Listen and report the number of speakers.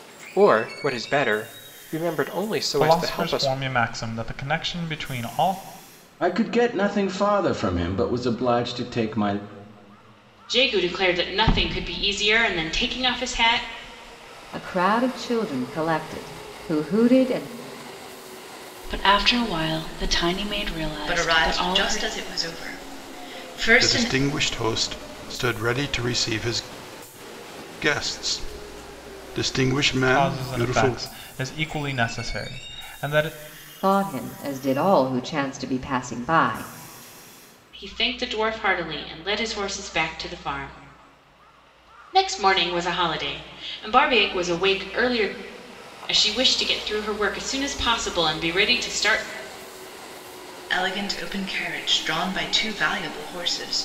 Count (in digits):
8